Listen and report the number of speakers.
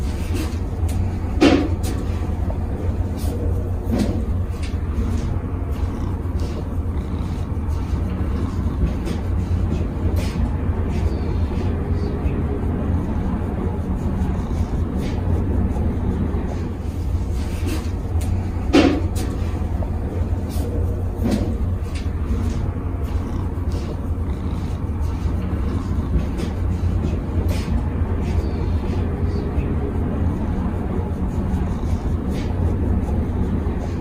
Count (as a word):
zero